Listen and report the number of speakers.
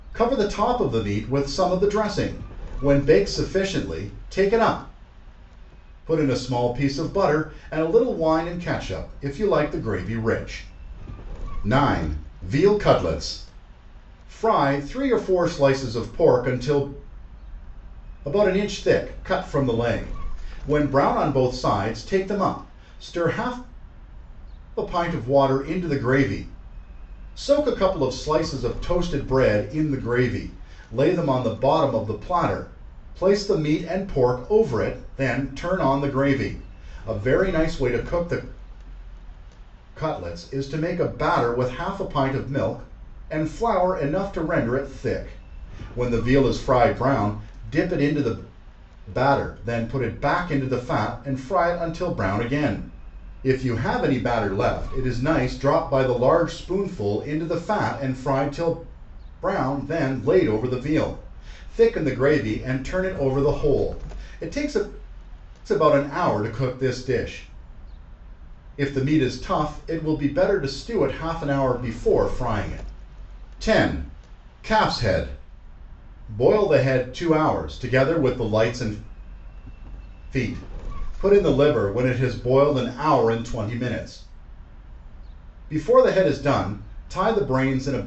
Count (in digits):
1